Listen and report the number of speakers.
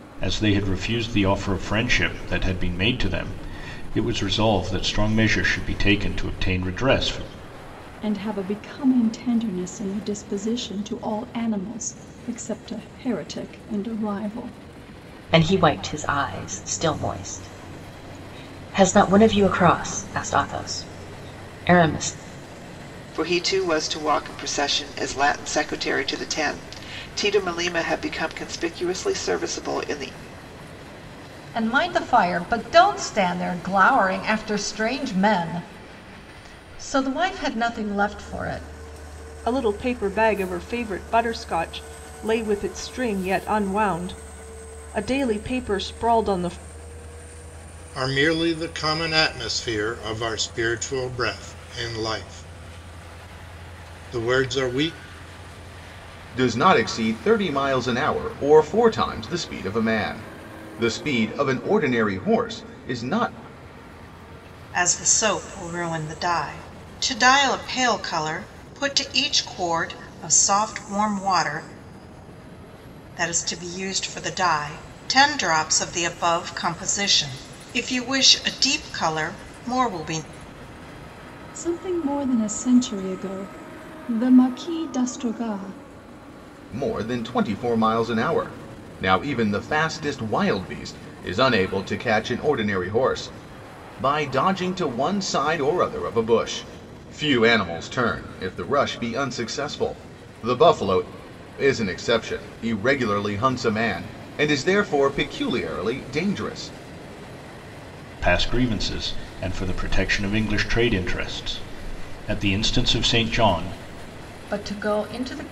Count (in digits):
9